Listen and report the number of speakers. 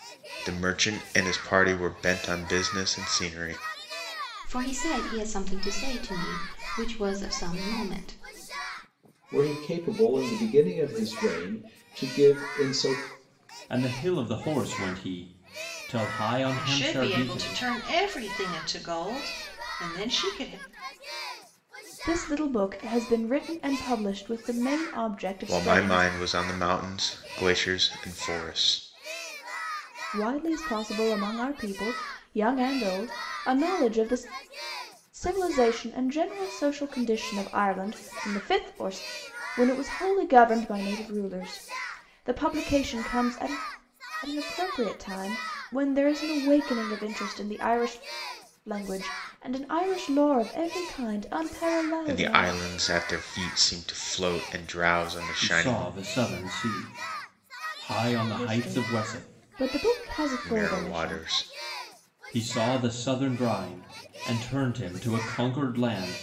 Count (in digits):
6